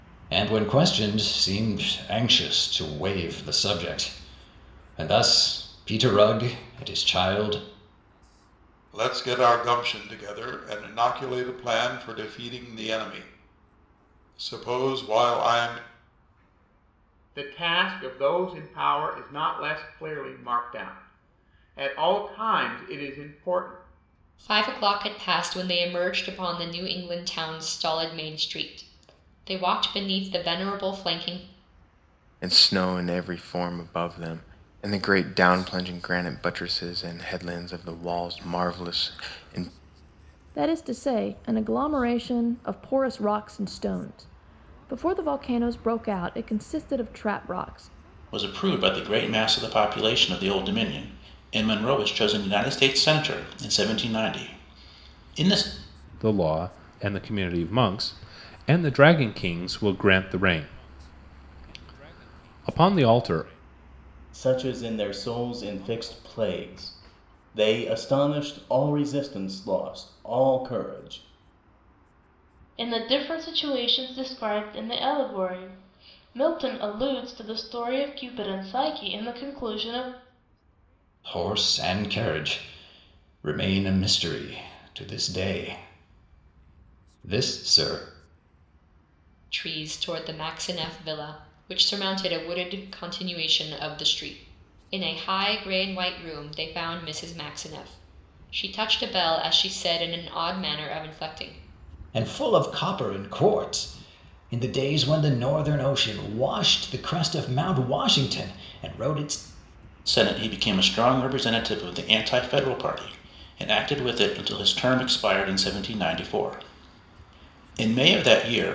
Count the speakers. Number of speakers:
10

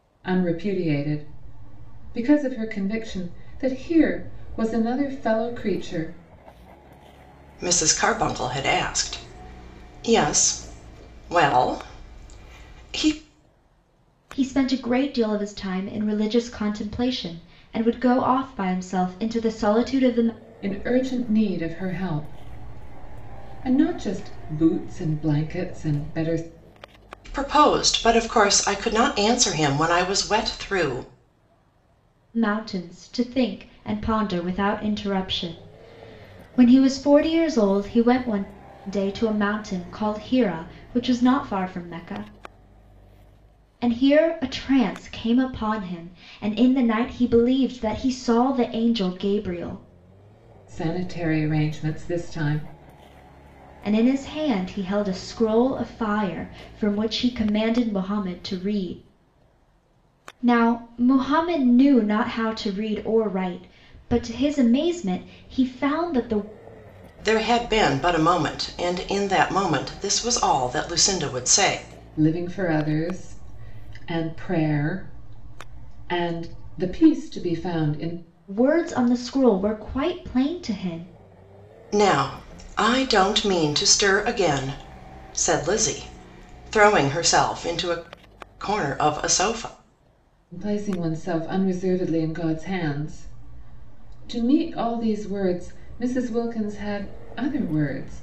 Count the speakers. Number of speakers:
3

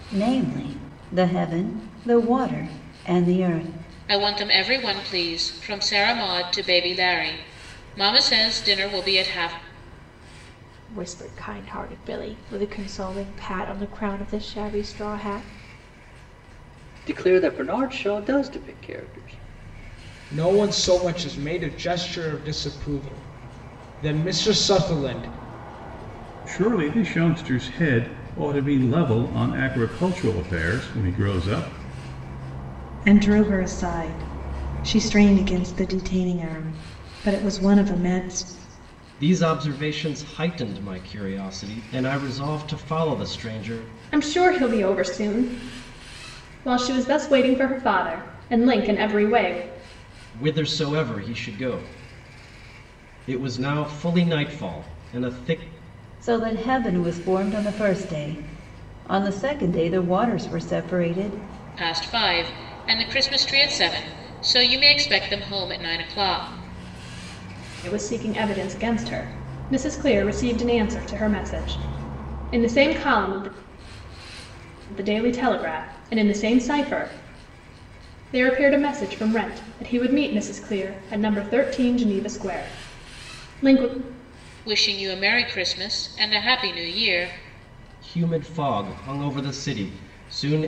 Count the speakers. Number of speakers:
9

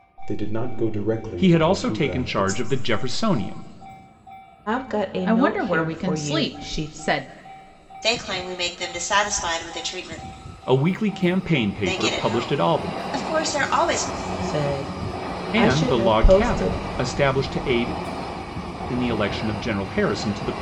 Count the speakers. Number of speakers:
5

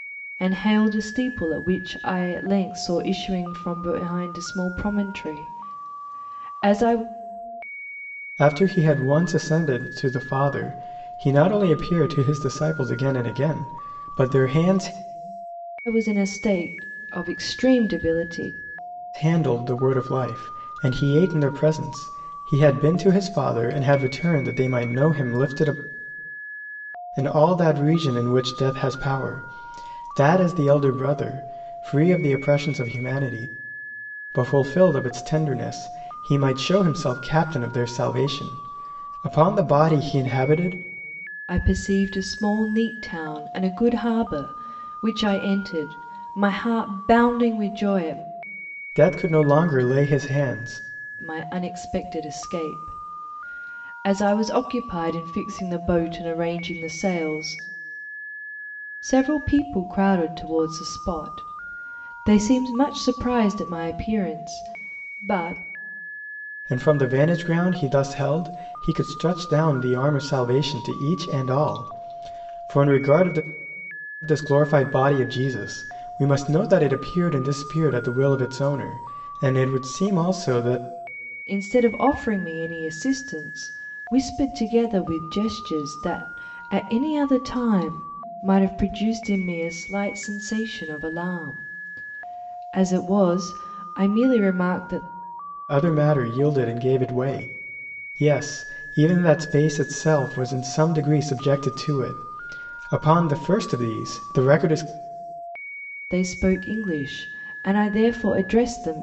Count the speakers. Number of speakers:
2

